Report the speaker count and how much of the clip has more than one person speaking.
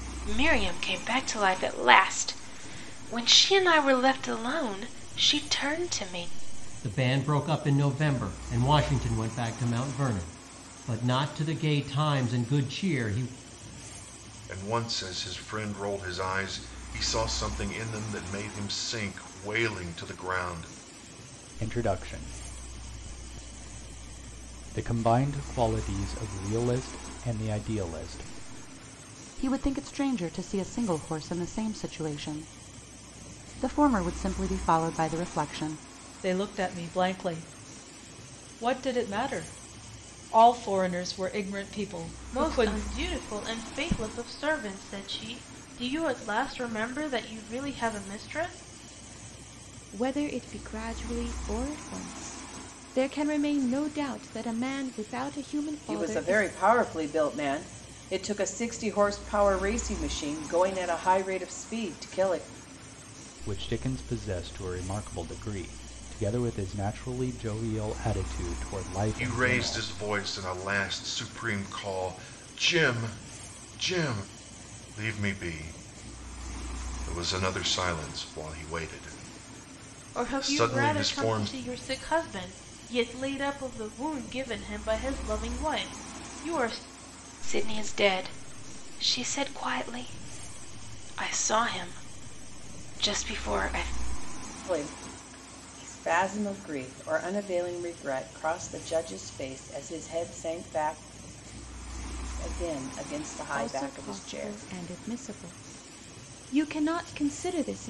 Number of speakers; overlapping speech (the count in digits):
9, about 4%